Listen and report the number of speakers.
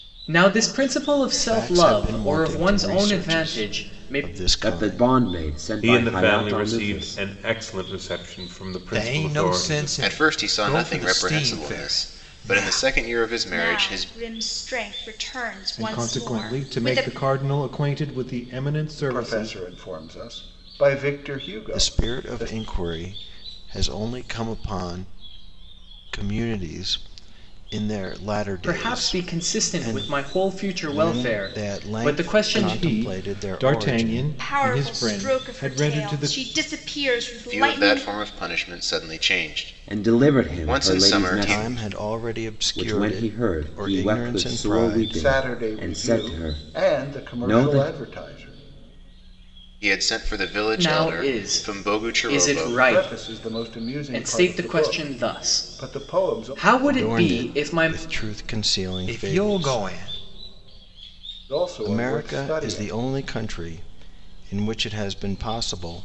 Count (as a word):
nine